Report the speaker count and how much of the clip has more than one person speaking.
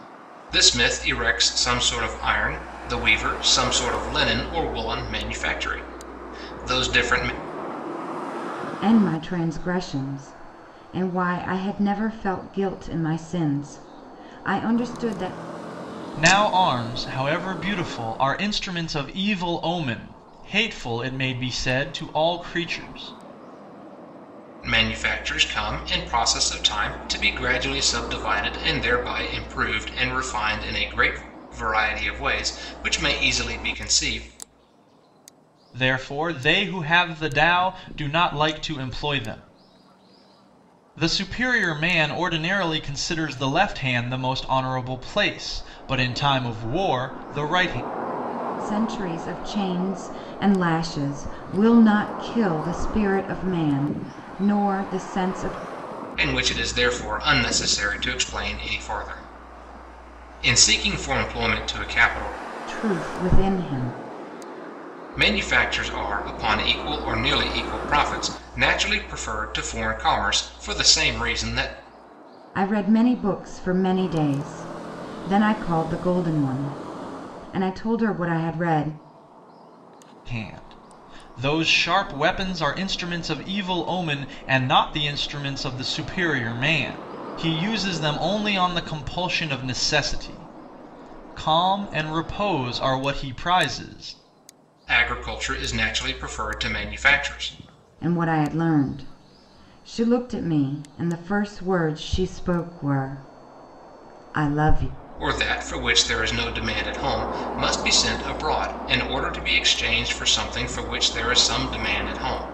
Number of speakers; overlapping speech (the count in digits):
3, no overlap